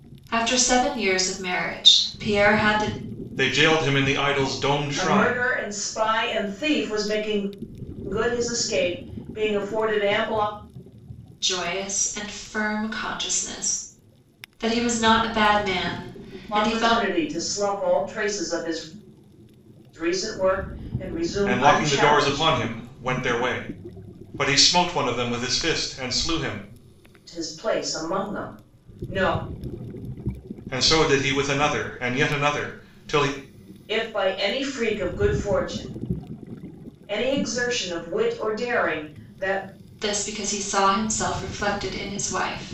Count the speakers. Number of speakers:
three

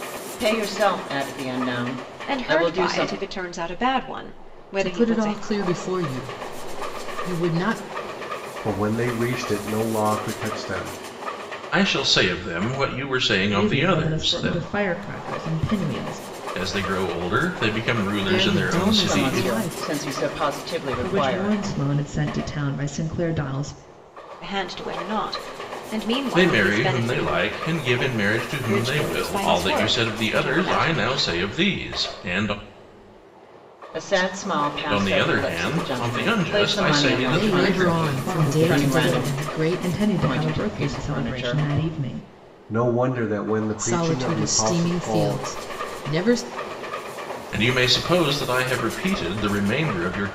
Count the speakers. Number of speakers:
six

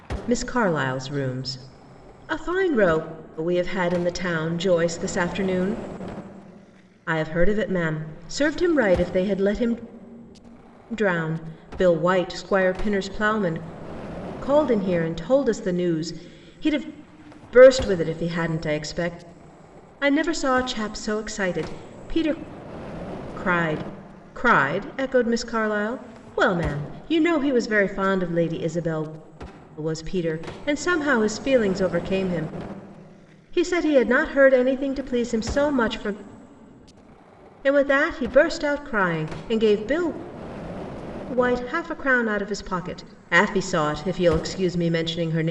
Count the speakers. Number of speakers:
one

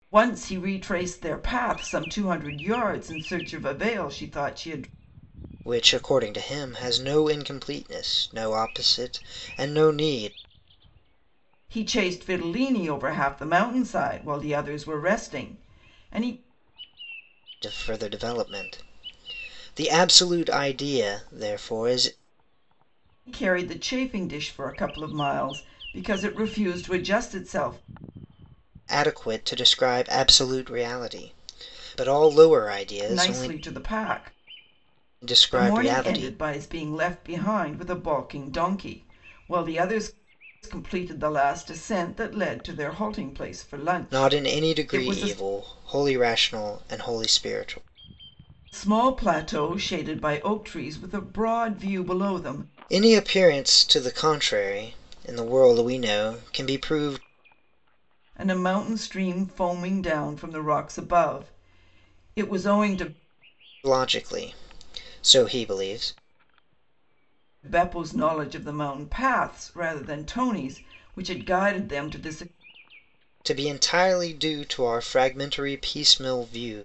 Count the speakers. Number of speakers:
two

